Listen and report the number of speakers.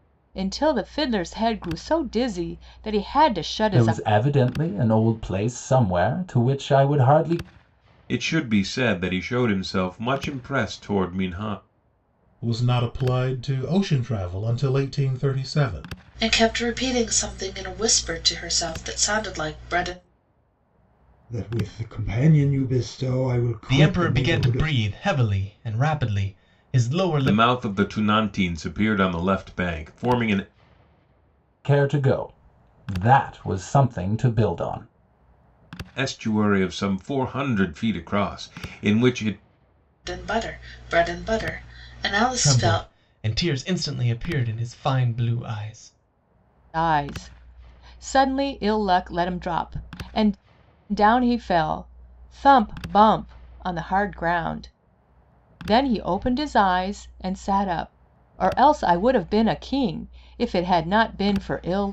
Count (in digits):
7